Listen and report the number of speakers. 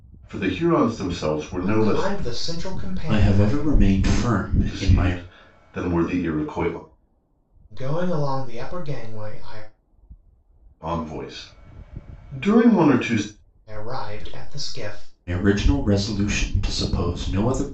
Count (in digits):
3